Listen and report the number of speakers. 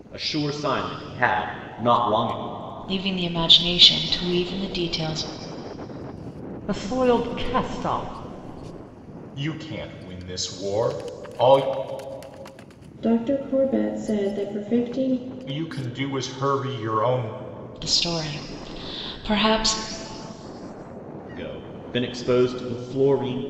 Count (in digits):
5